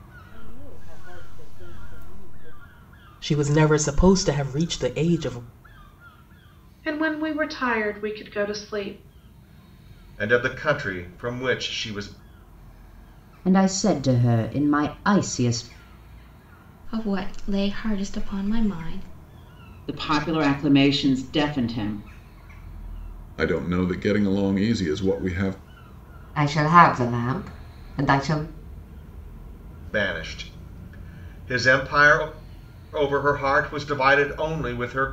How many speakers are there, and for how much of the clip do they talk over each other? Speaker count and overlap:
9, no overlap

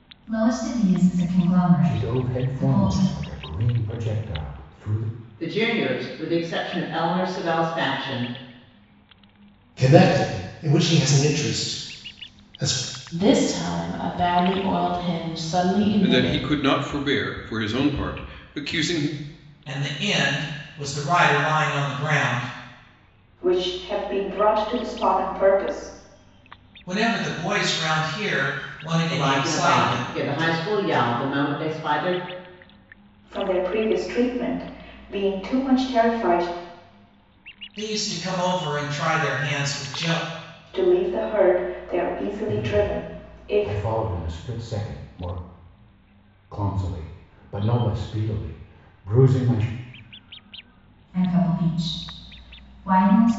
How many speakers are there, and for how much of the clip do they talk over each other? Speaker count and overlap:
8, about 8%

